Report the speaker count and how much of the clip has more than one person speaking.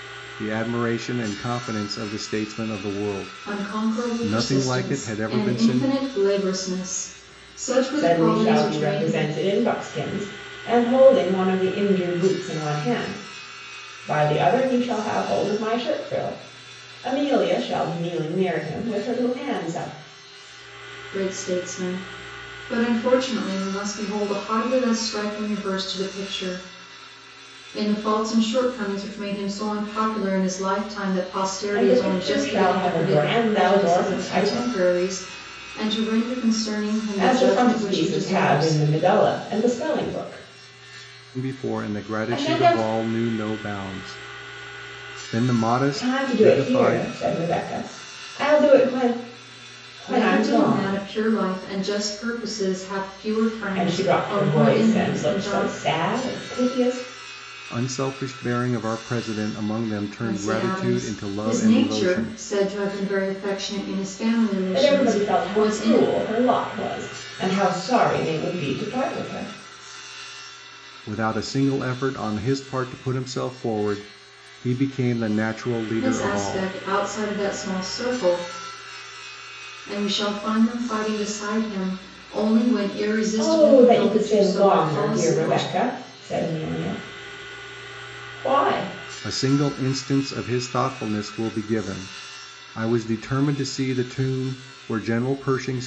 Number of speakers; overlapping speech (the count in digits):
3, about 22%